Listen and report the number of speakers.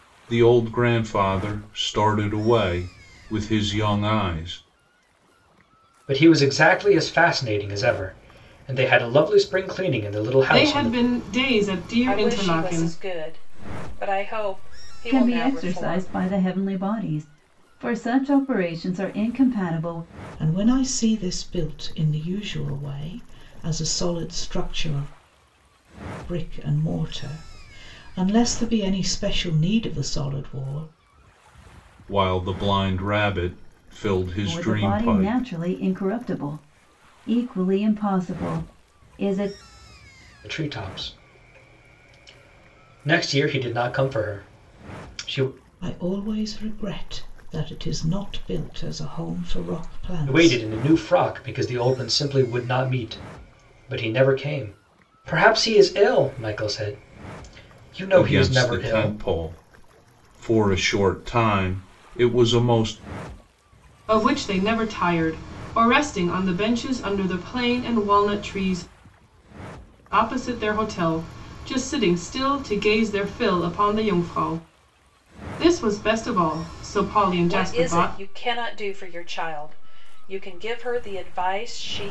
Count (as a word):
six